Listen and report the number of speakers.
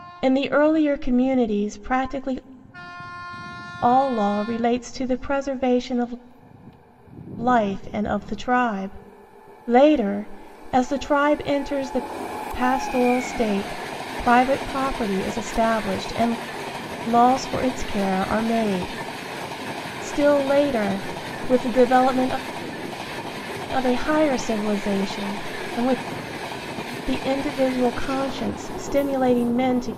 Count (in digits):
1